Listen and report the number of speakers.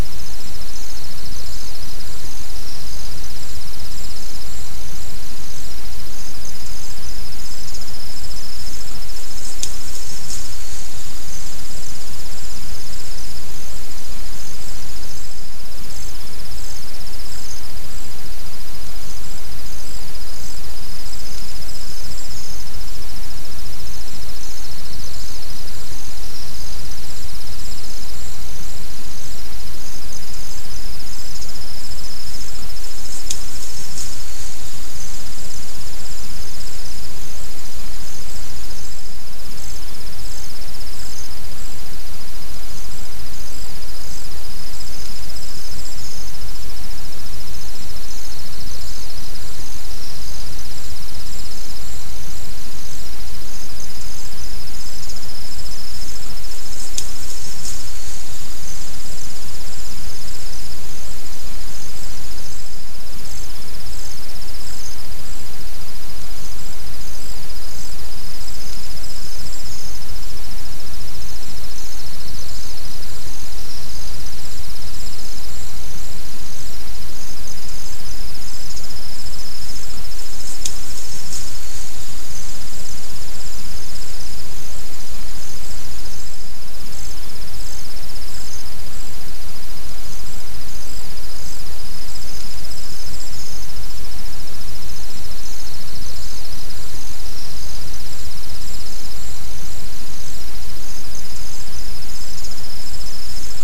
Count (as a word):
zero